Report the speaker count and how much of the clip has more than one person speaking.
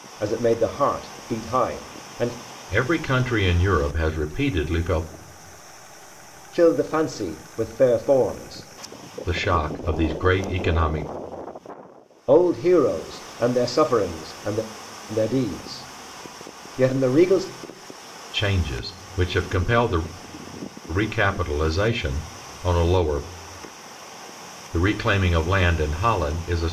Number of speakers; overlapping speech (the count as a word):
two, no overlap